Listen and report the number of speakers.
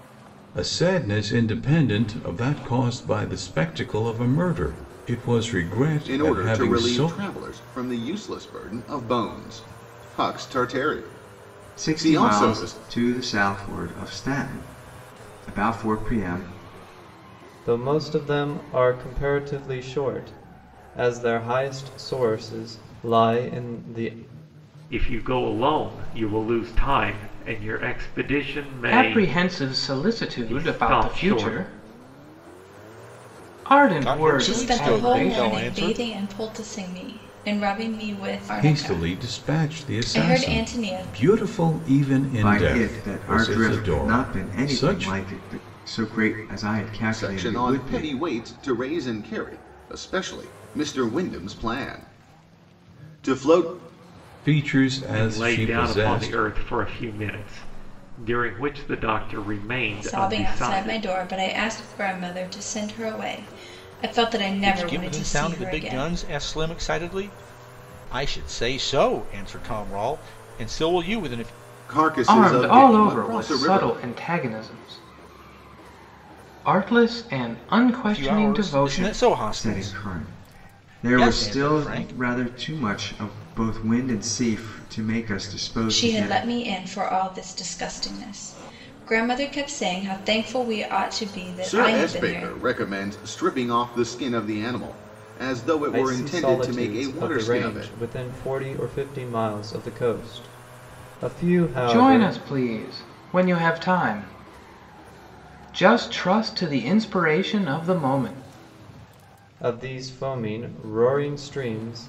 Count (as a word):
eight